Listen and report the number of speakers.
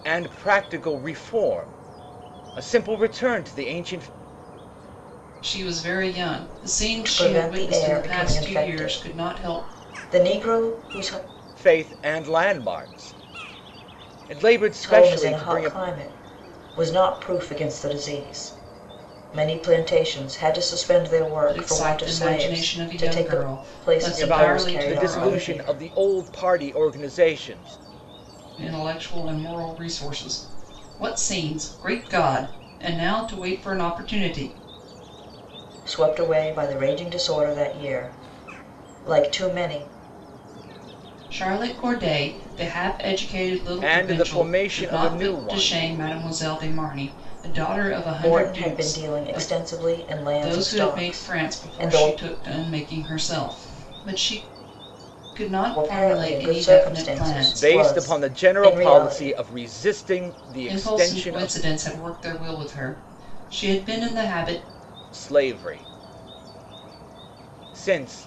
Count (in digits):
3